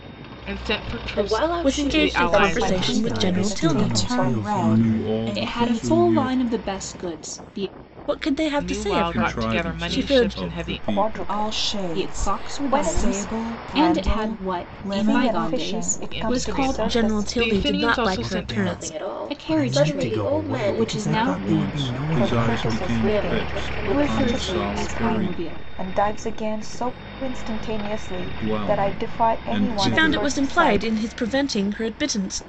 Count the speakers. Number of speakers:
eight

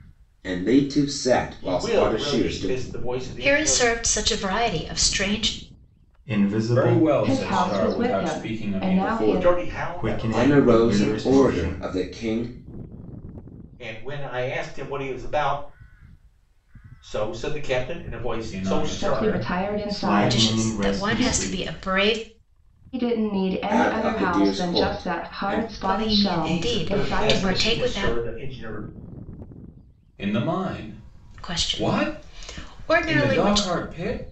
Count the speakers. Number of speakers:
six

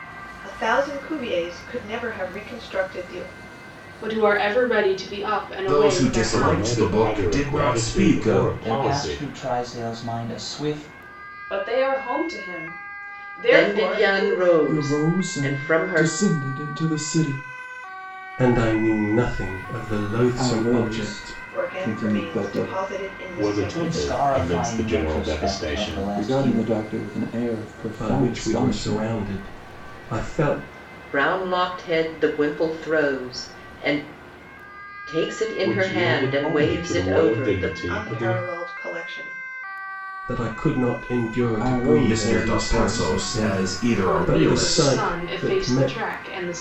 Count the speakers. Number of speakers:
nine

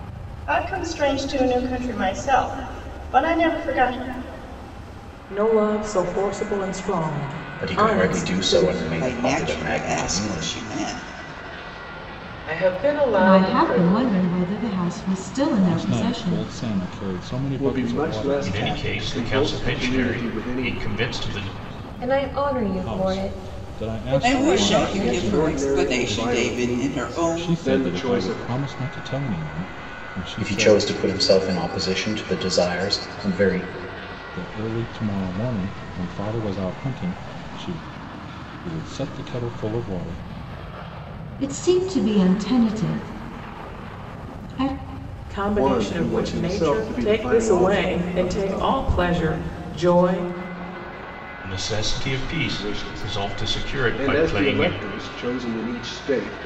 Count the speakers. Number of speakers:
ten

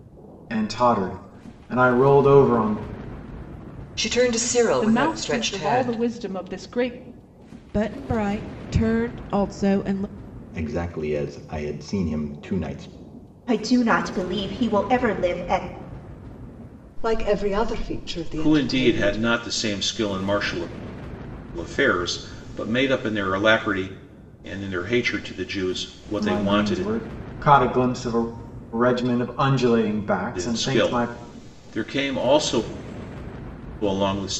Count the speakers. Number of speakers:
eight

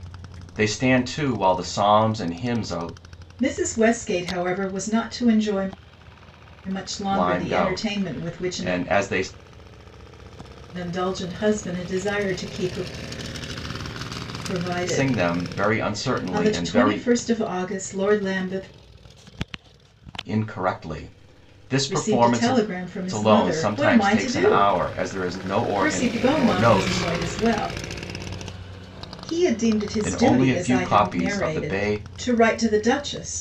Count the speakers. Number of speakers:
two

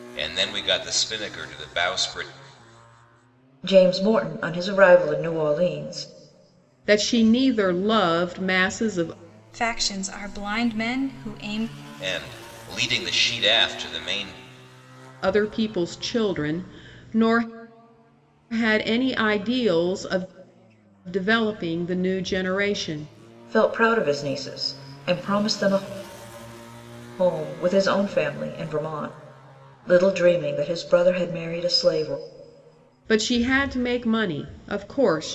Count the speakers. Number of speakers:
four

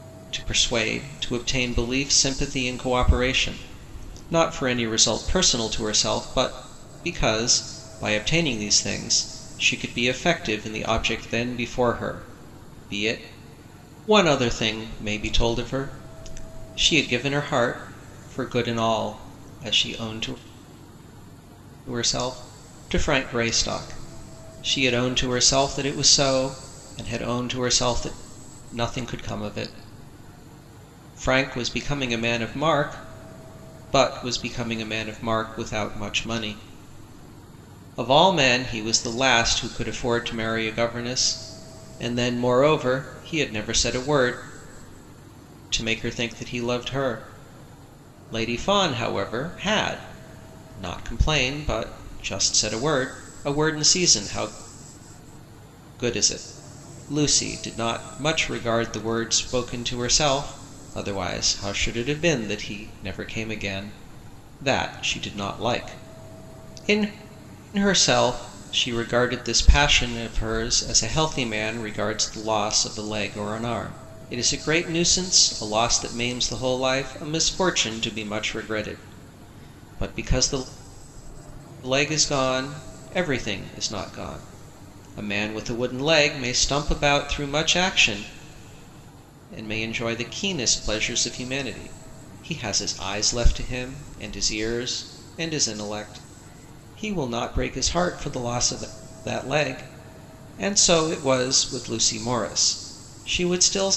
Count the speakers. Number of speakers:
one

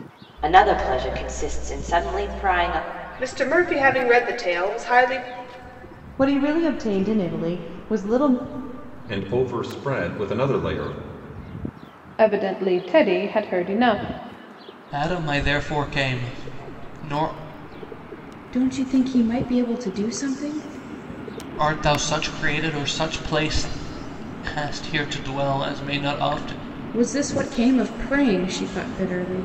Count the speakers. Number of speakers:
seven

